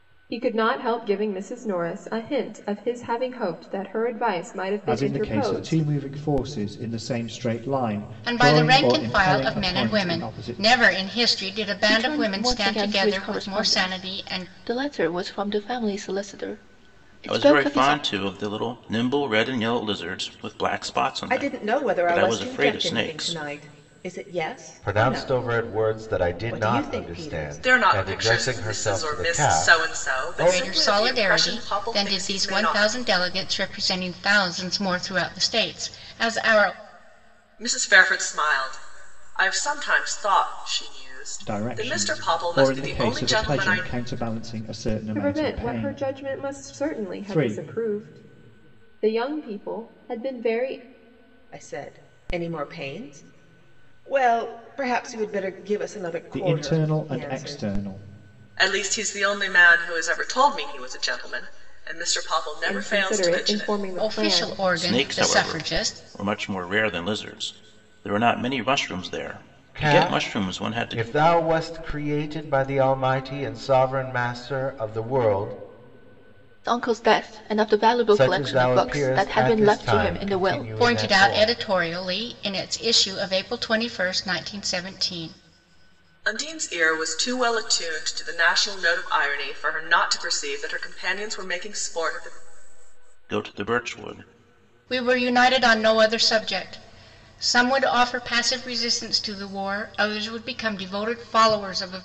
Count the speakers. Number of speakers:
8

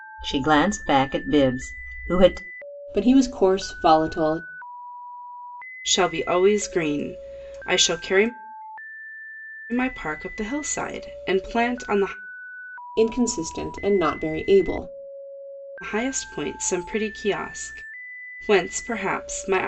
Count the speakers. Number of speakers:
3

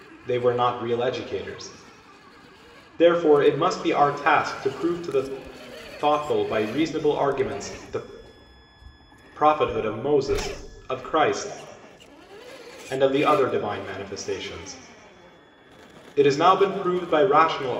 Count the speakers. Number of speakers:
1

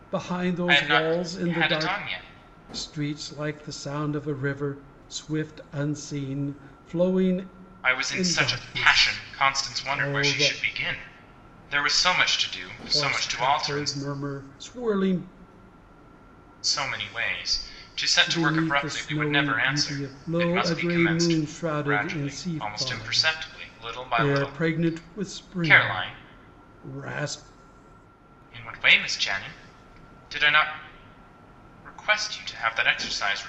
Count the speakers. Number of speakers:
2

